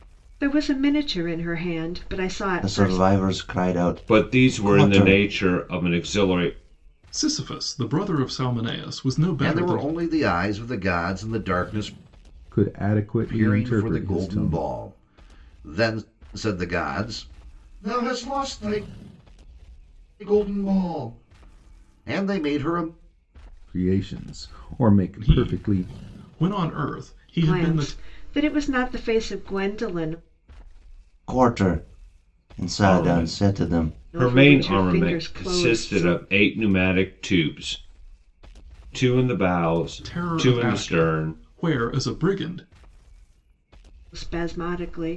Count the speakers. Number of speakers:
six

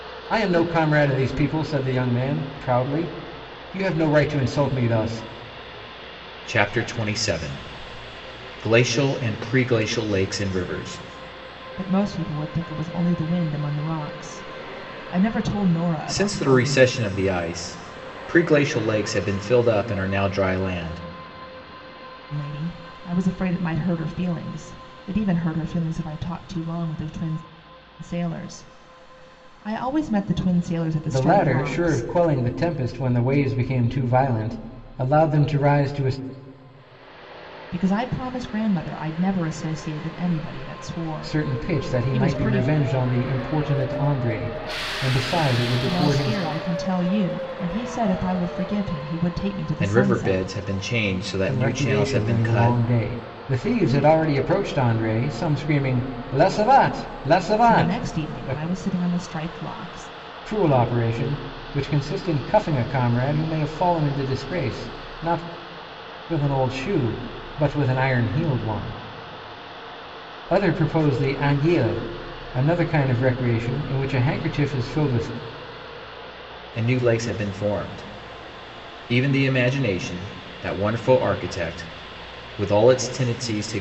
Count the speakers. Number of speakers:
three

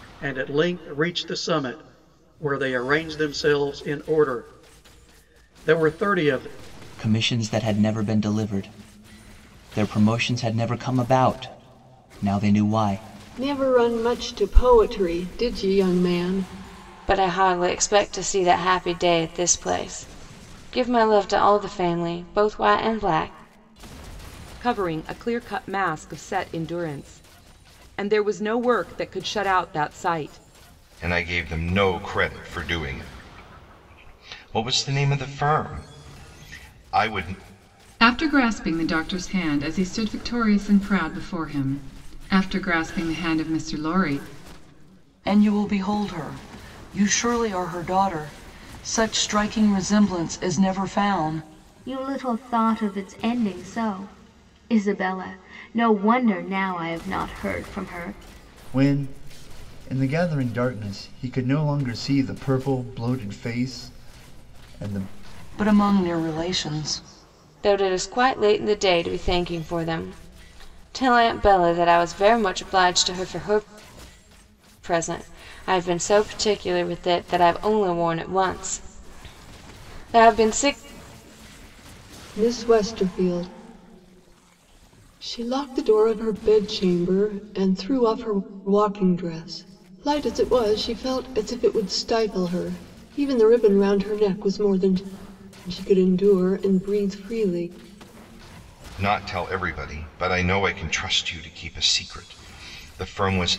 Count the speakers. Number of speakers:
ten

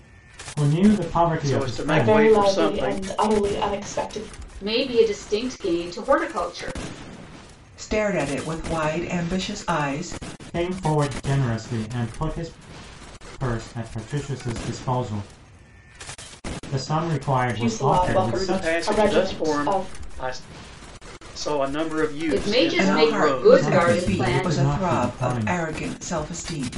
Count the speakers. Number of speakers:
five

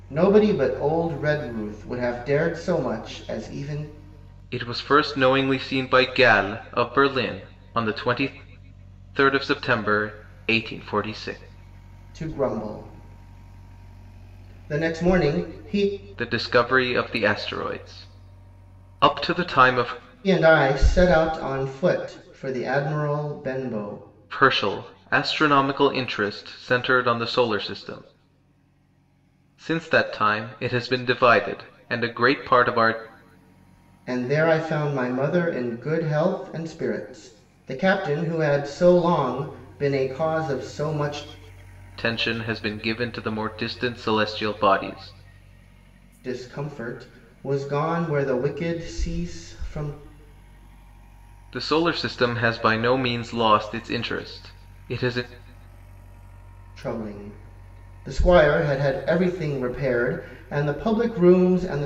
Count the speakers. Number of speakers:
two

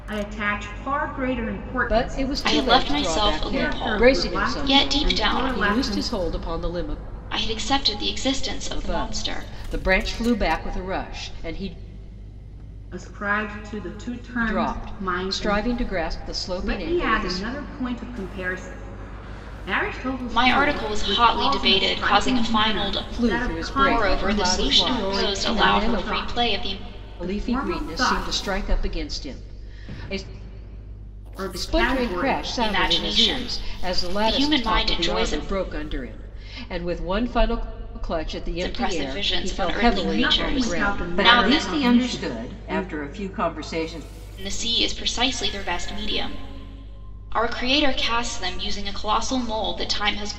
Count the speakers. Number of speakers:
three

